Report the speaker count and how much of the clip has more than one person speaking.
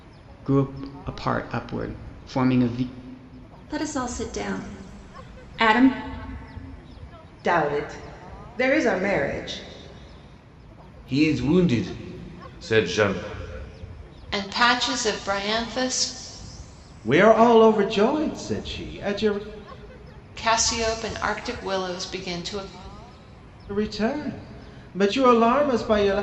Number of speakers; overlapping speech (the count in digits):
6, no overlap